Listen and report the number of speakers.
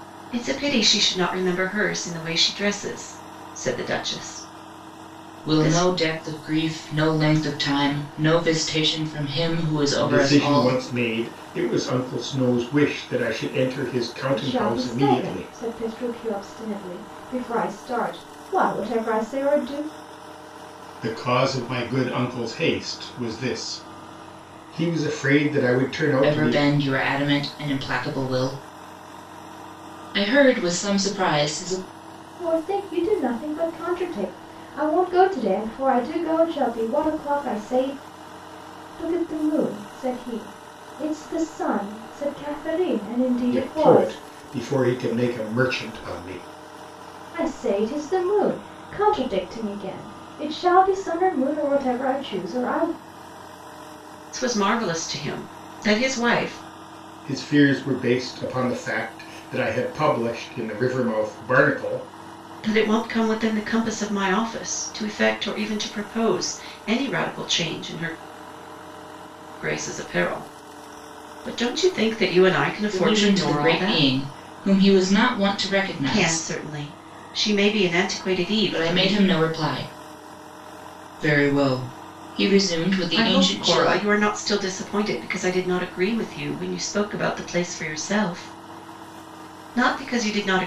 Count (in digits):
4